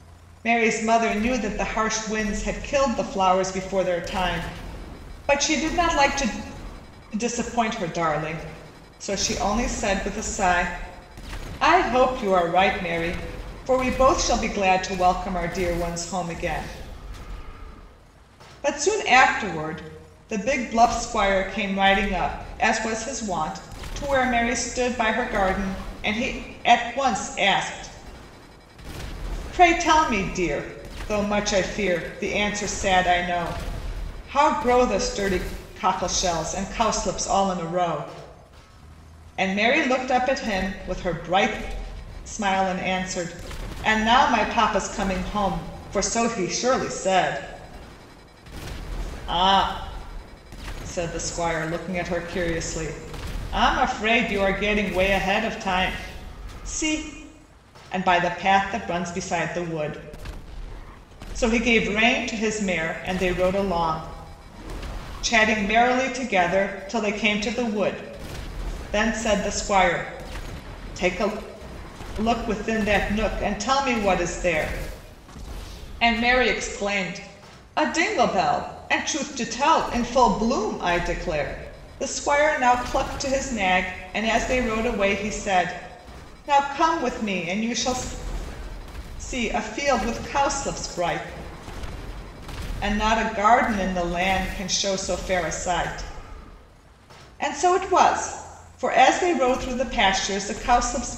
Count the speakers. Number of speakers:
one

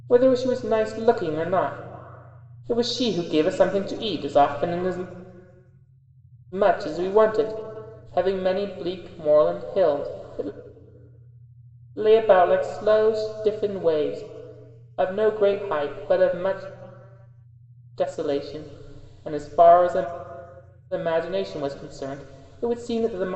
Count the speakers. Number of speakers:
one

